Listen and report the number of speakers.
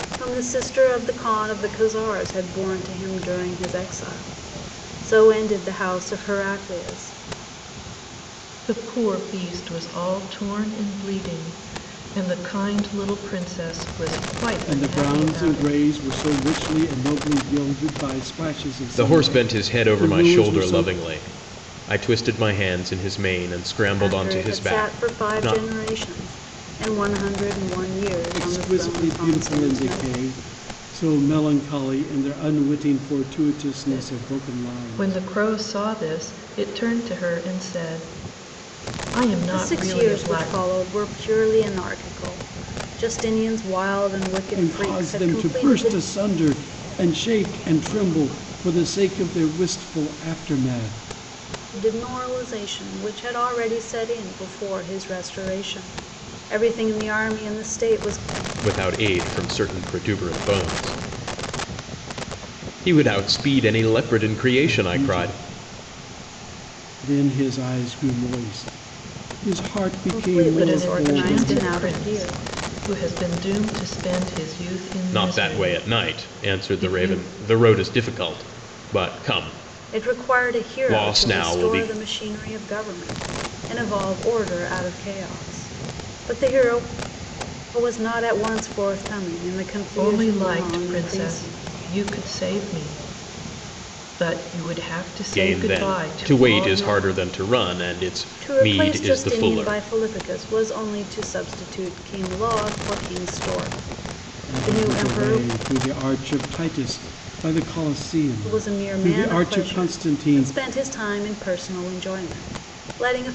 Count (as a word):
four